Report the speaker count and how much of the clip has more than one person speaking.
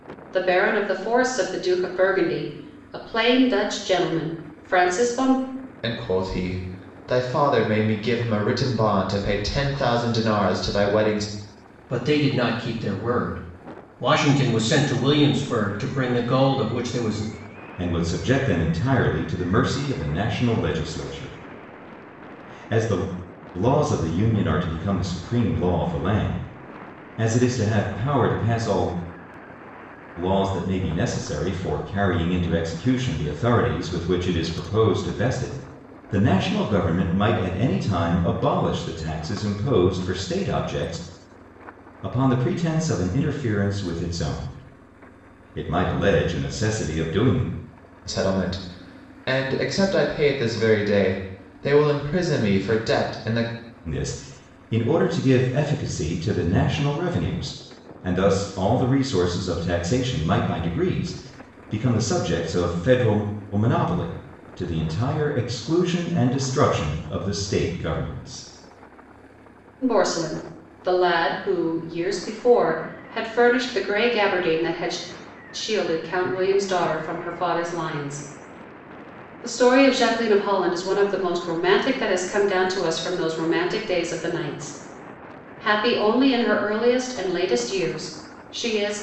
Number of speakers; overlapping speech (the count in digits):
4, no overlap